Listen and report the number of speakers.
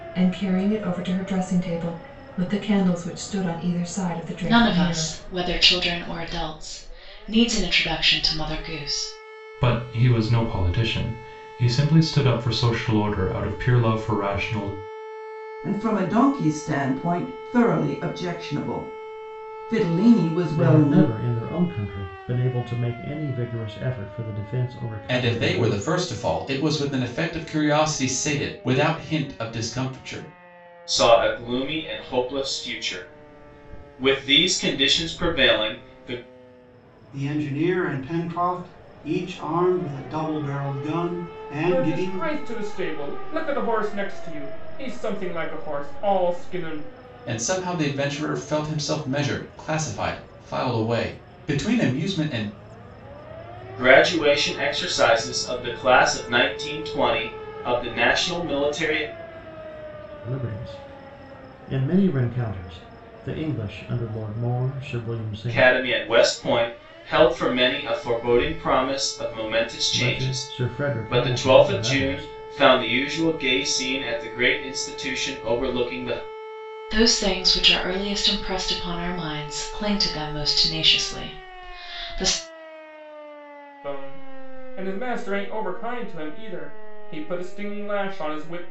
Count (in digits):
9